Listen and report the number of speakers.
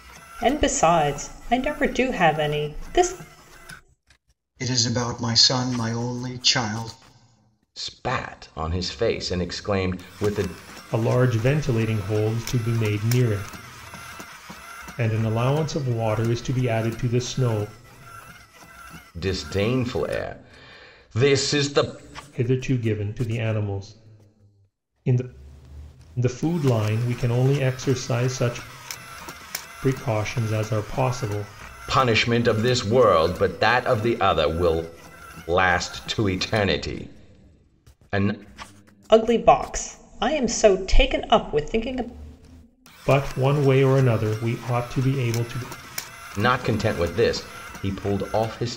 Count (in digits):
4